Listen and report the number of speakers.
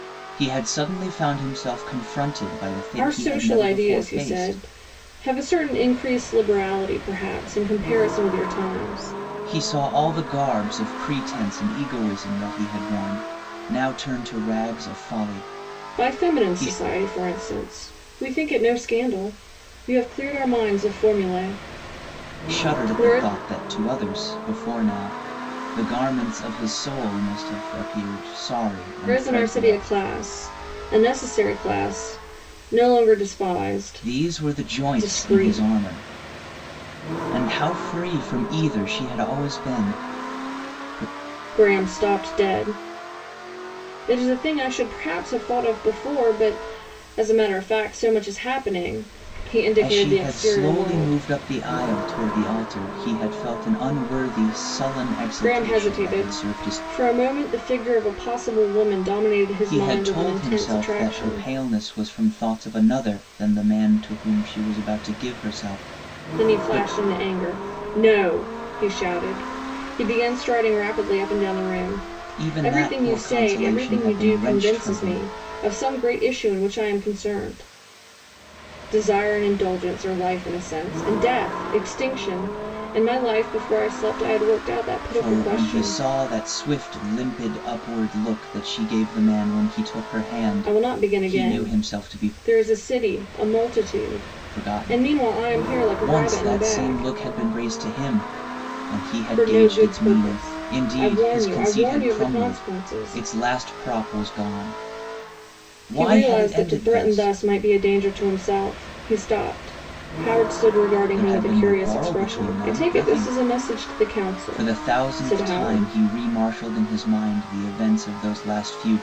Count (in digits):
2